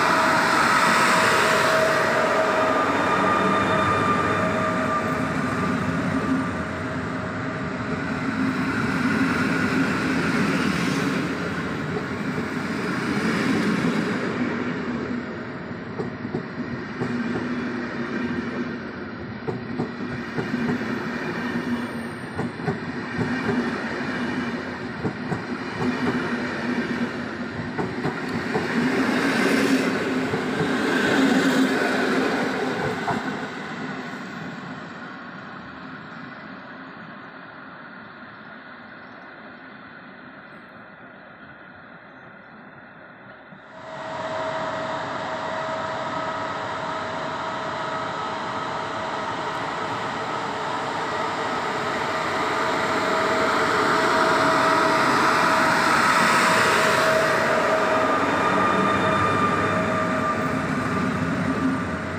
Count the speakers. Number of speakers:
zero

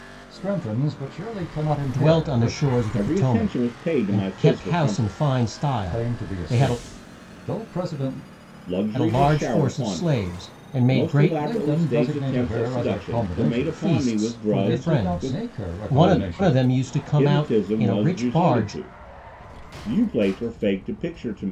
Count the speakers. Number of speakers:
three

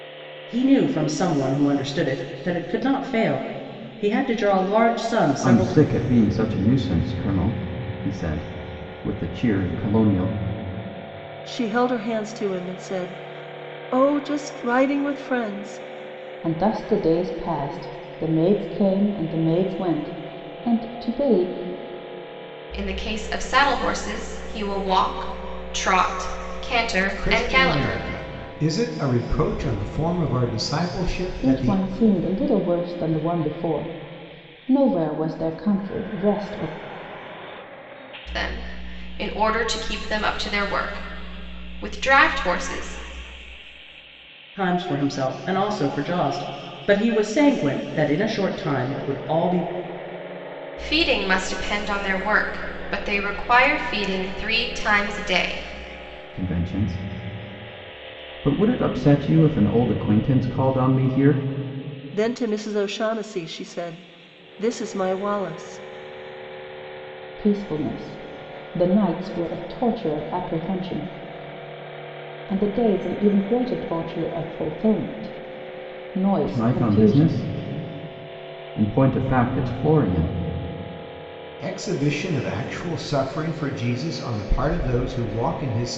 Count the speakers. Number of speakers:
six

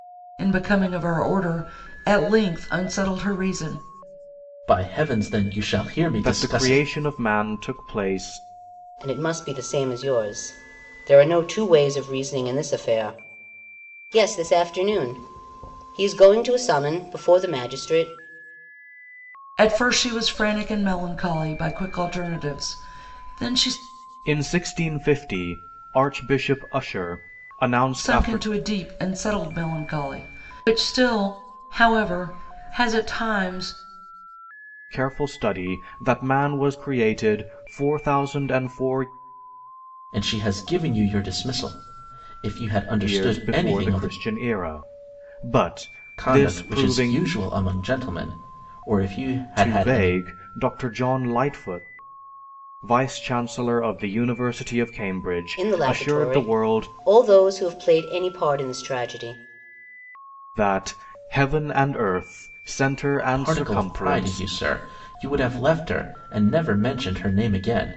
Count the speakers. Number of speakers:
four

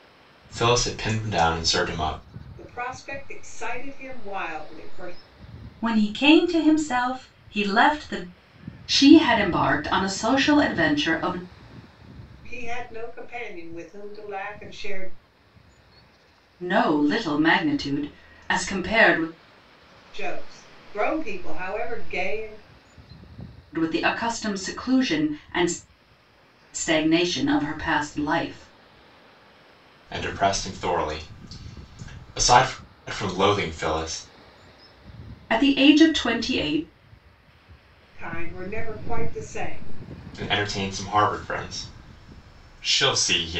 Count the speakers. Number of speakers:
three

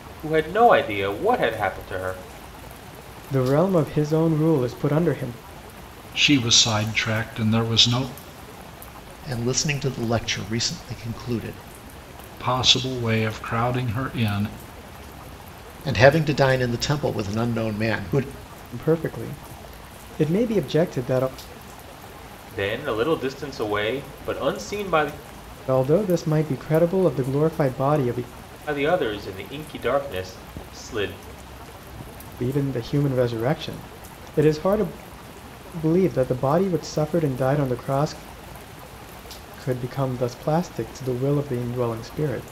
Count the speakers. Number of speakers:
four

